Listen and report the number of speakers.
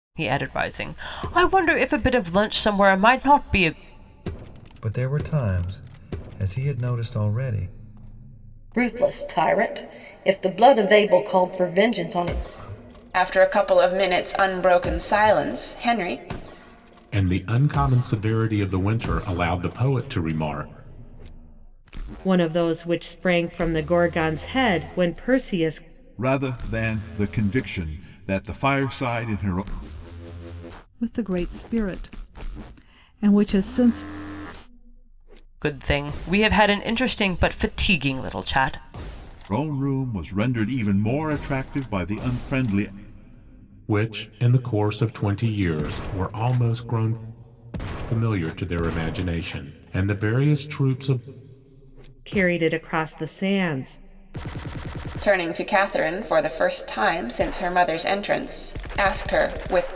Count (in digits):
8